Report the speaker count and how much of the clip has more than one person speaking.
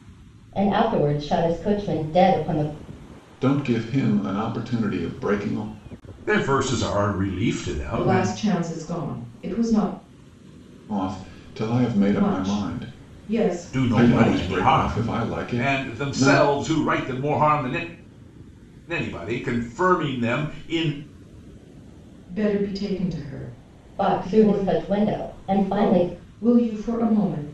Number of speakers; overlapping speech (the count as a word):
four, about 18%